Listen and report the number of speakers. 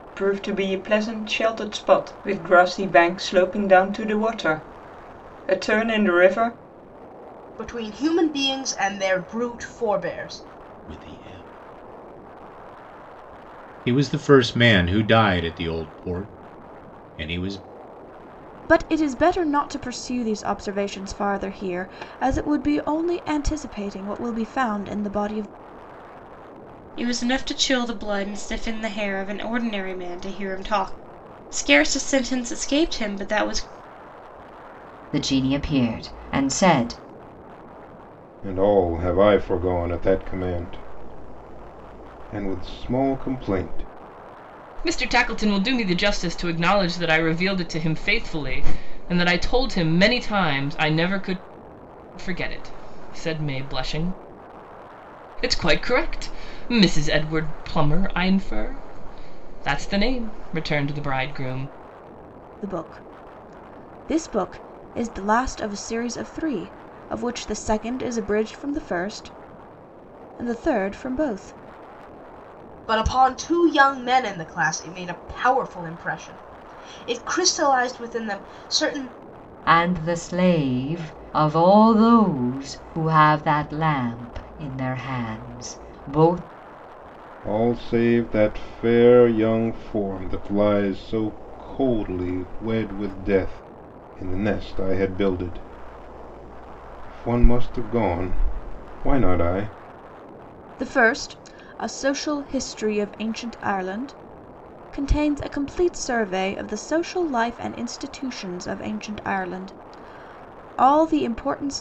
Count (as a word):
eight